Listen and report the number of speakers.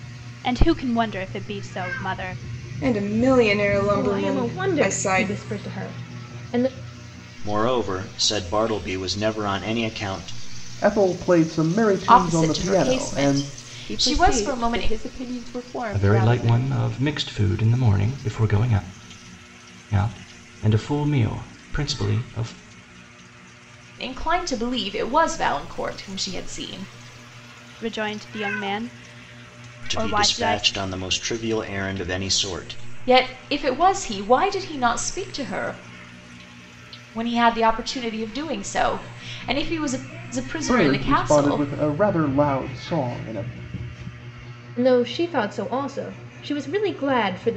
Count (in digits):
8